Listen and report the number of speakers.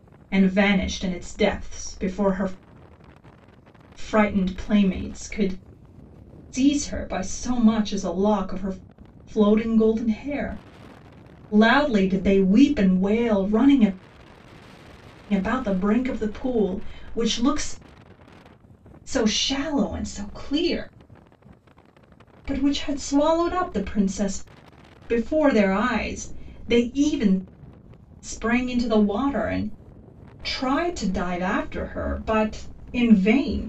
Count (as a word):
one